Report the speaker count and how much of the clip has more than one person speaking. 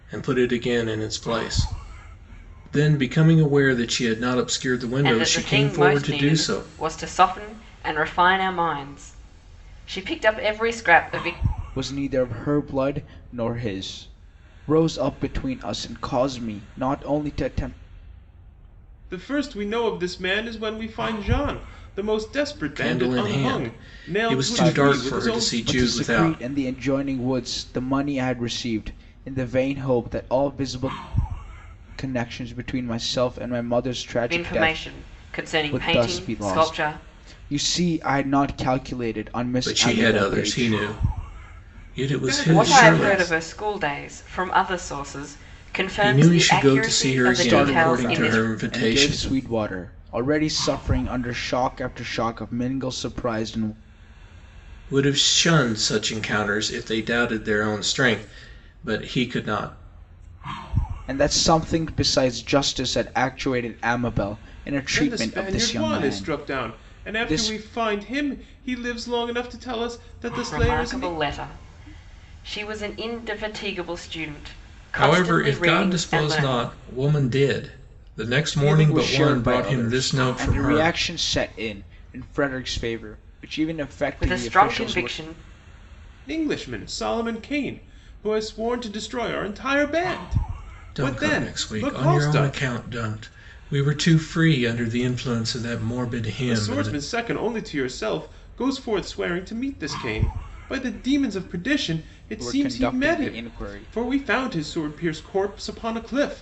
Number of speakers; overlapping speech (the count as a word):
four, about 24%